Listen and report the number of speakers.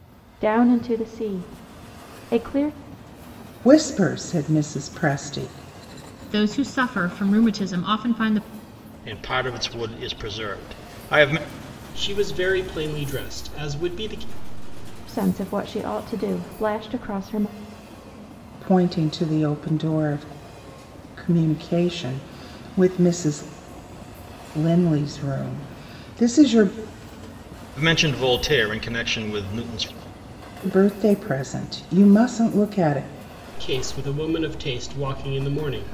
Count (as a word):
five